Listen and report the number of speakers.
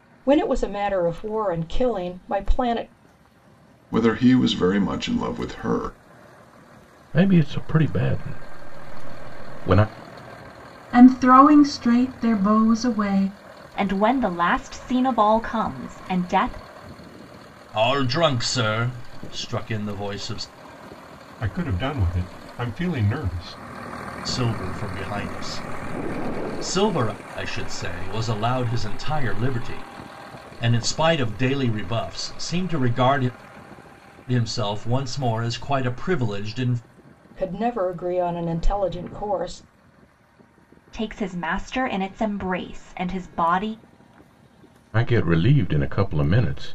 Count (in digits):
7